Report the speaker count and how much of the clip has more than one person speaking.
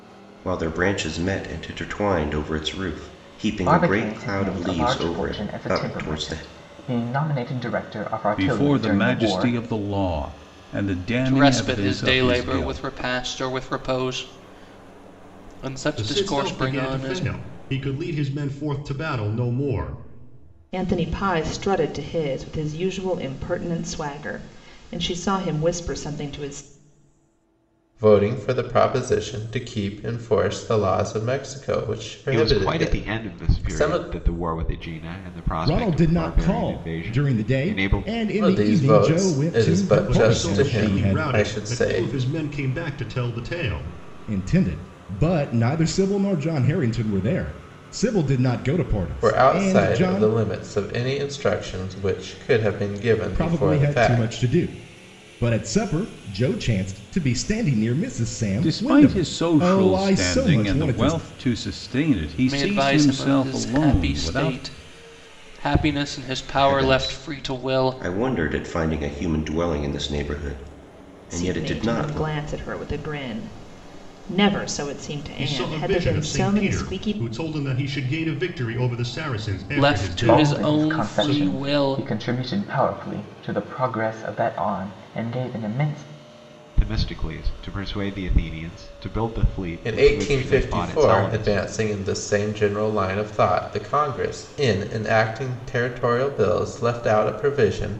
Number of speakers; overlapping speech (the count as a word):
nine, about 31%